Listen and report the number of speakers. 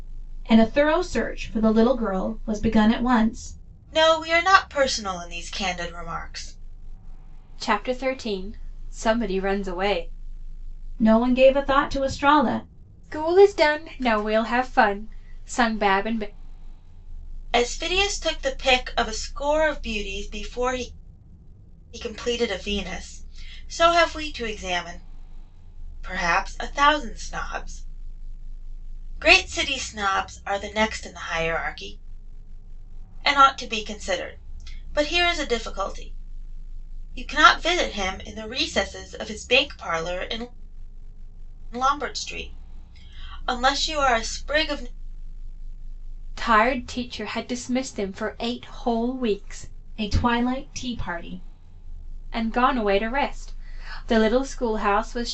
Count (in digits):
3